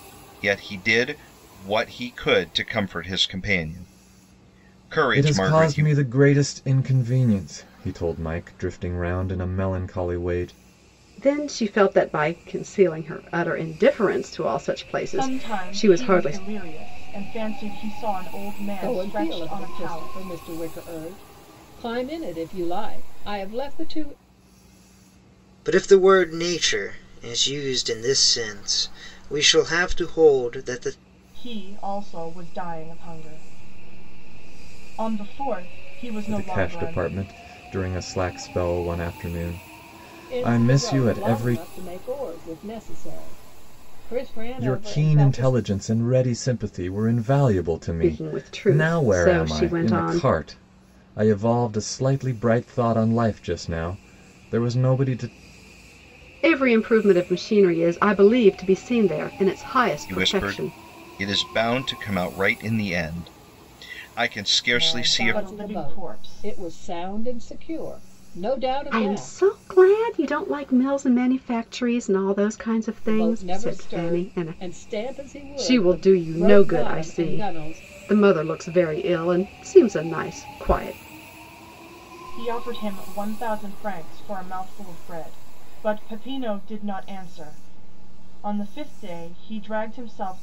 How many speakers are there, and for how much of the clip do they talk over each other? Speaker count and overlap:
6, about 18%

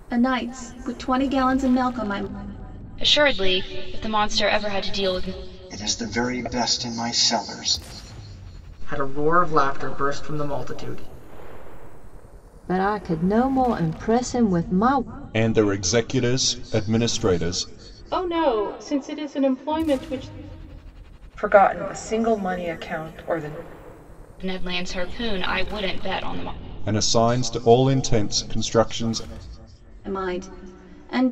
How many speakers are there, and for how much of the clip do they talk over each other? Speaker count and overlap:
8, no overlap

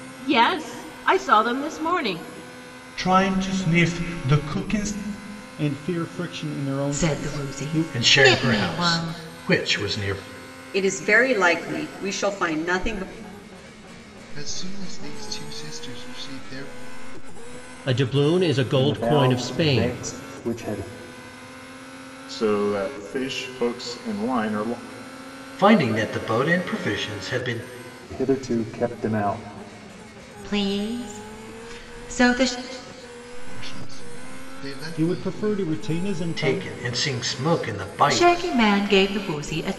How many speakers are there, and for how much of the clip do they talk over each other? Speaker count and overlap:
10, about 12%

